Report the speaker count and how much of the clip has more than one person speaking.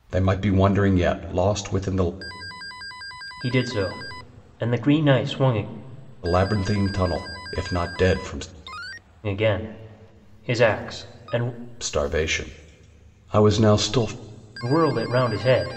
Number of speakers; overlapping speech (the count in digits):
2, no overlap